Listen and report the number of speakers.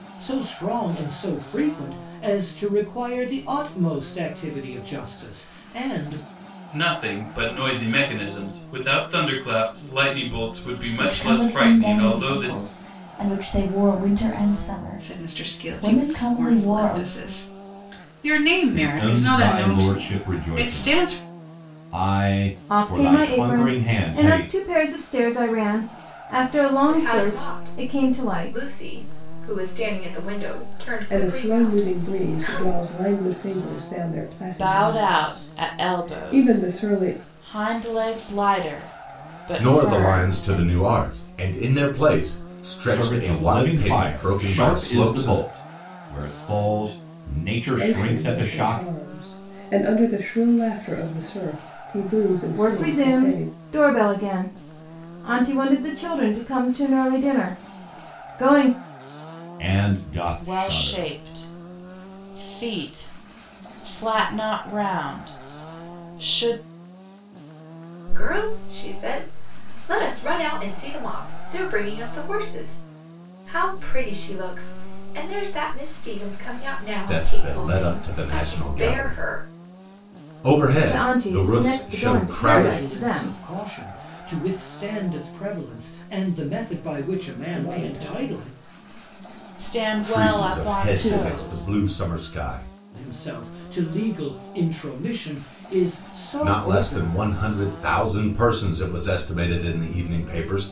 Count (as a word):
ten